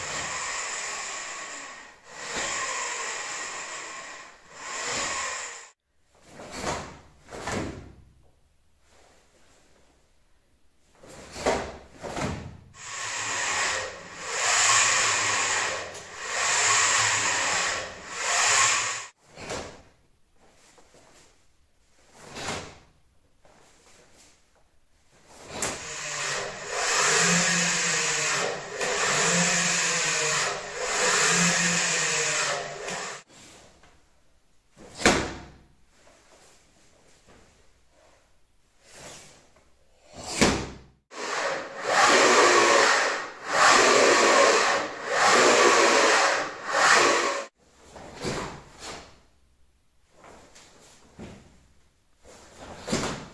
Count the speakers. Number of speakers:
0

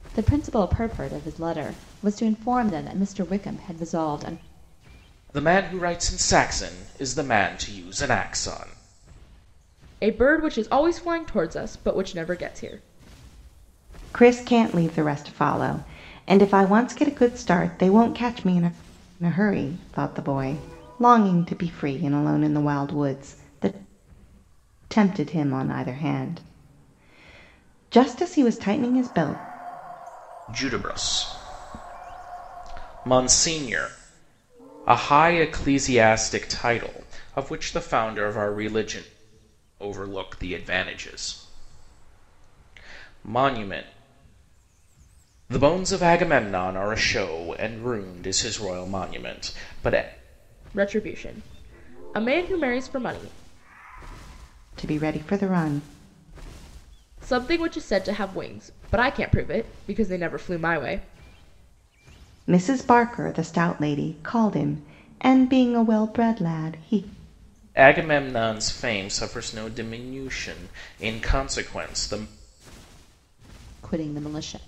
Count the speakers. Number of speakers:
4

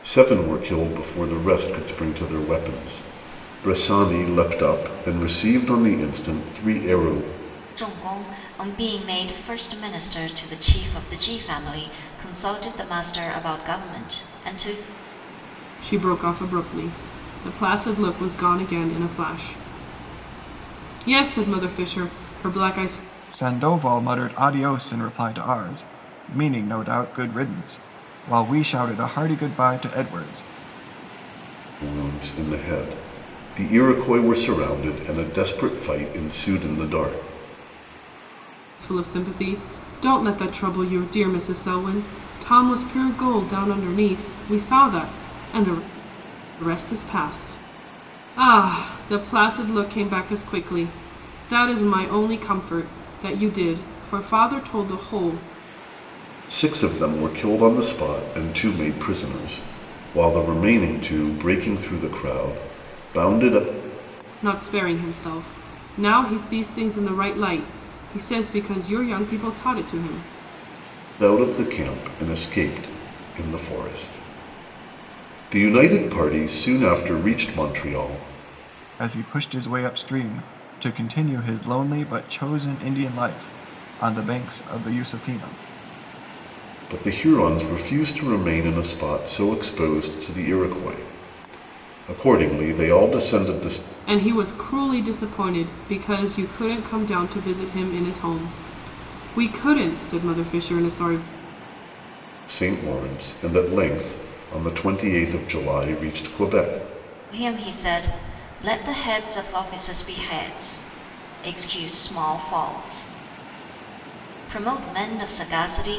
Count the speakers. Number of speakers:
4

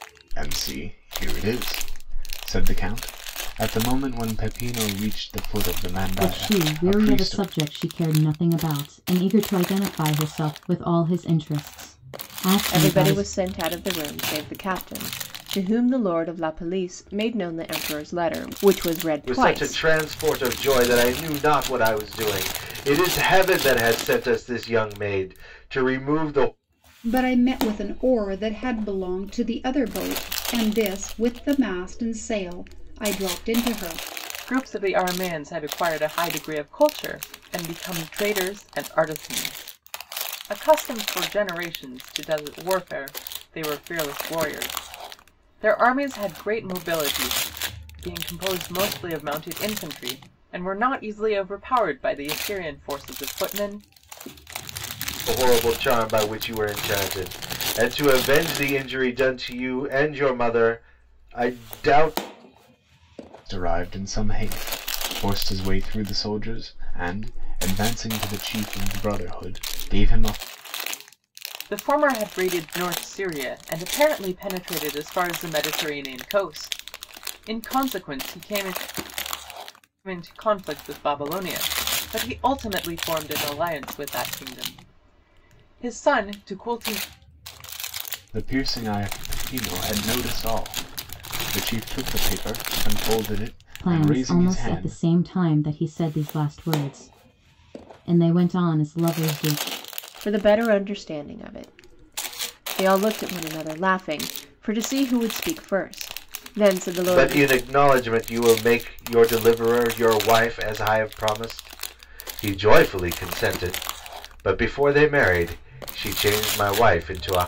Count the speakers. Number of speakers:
6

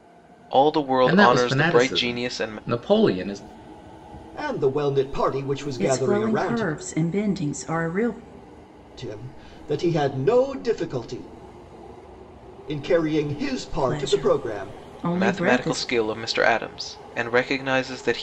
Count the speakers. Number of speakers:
4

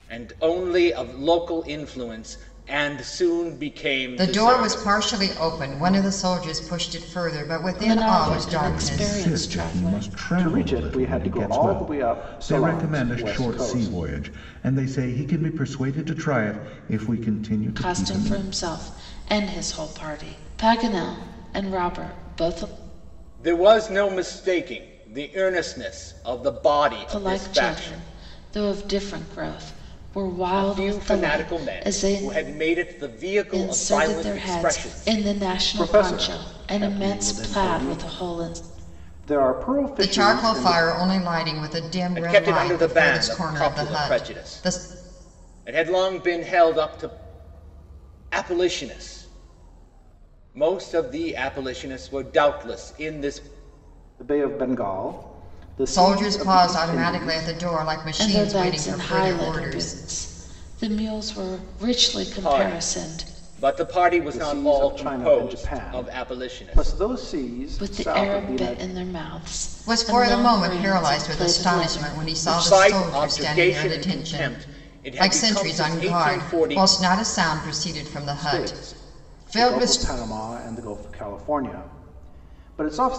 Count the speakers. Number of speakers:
5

